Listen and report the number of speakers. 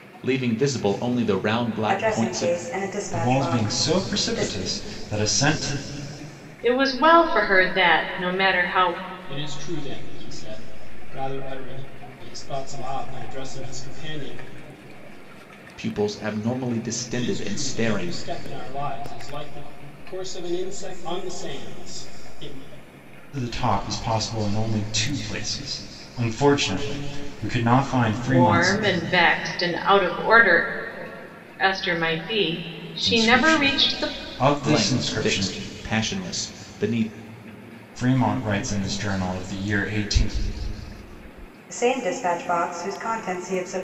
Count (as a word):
five